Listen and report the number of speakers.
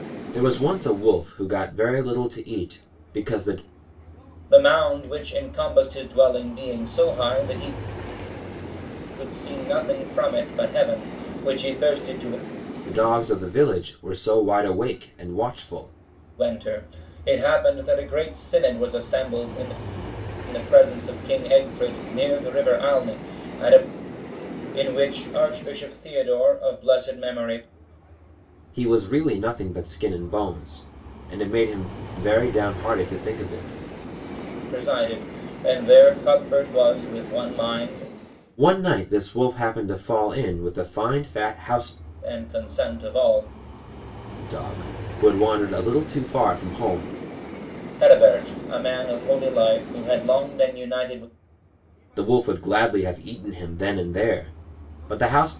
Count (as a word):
two